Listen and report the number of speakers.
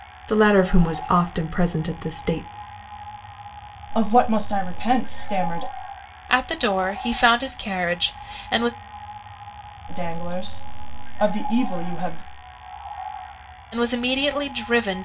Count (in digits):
3